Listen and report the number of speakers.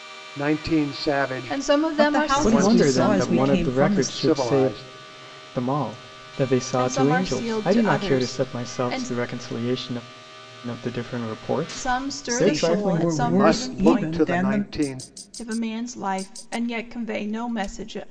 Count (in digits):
4